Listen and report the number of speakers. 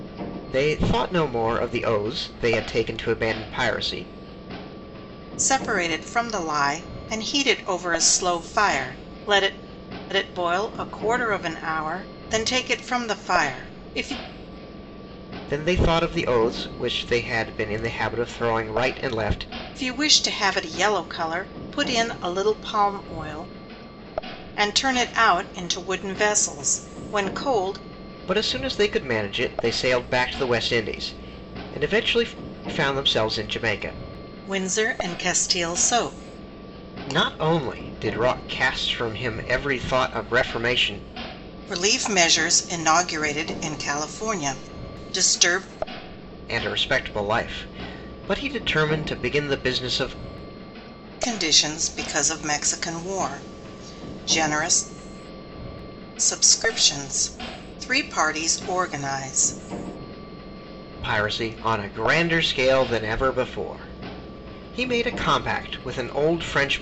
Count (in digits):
2